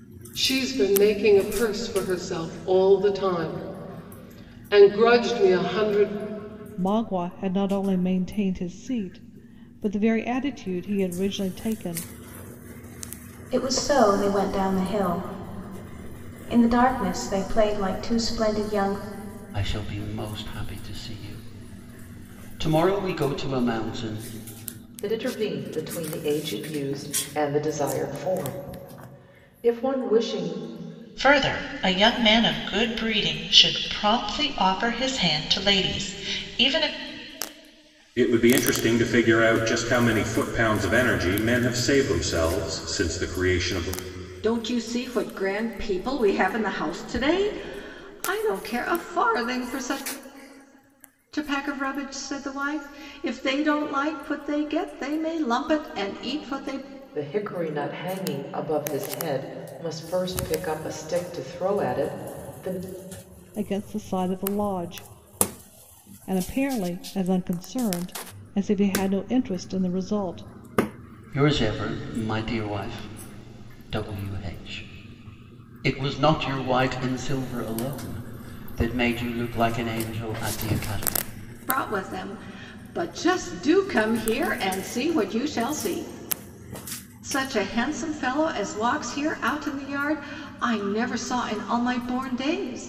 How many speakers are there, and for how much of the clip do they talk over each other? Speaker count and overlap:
8, no overlap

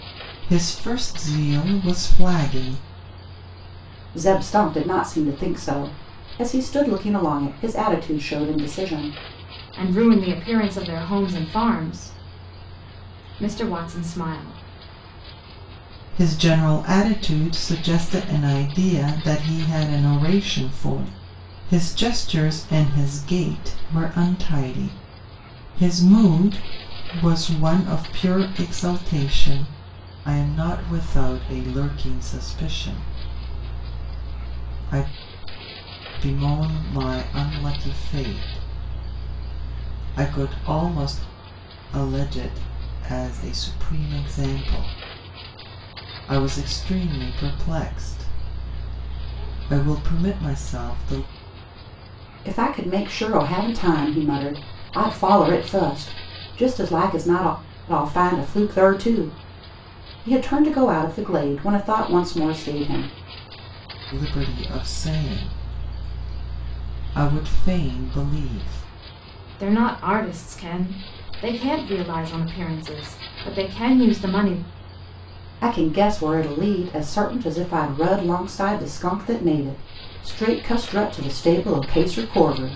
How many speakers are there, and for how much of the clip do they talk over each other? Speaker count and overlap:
3, no overlap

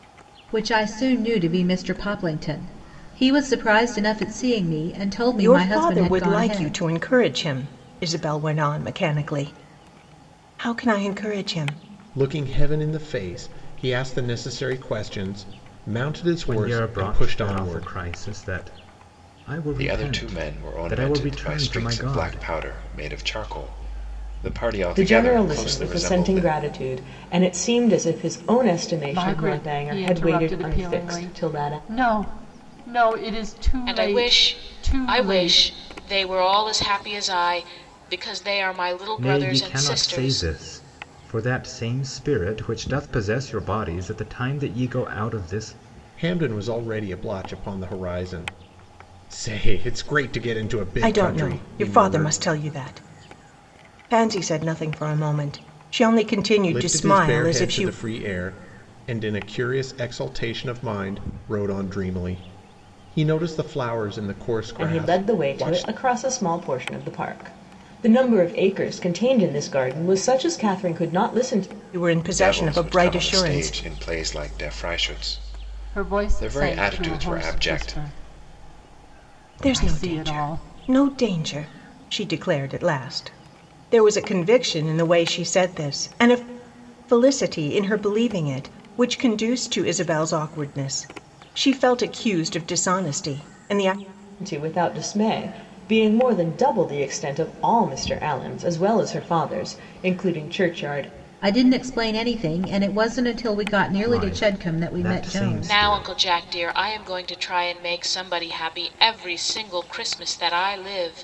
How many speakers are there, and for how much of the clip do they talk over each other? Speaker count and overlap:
8, about 22%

